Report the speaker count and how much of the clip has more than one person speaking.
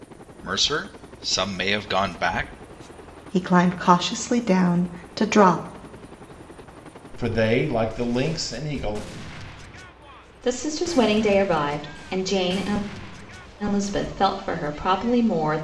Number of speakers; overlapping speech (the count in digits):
4, no overlap